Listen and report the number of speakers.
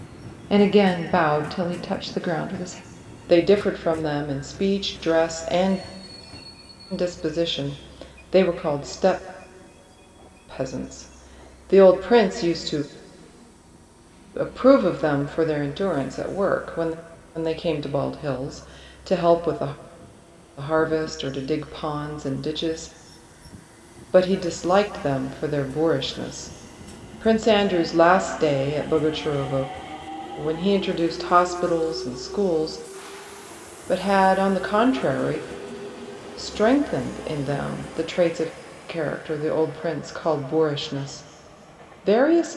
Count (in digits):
1